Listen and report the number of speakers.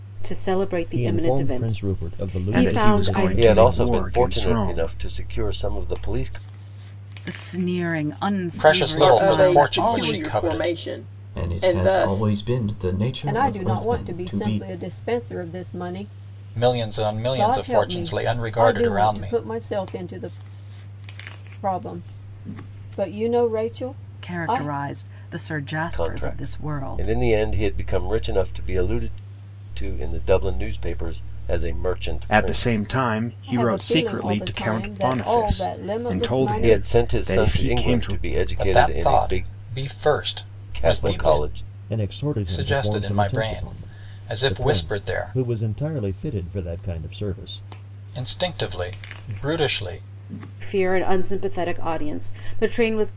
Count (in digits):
9